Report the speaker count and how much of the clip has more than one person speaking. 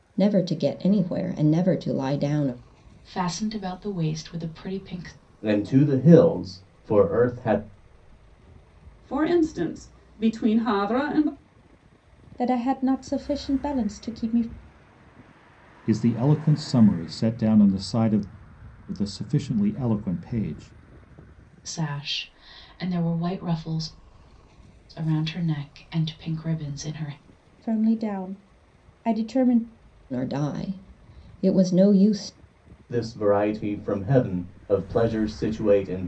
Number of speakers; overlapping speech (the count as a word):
six, no overlap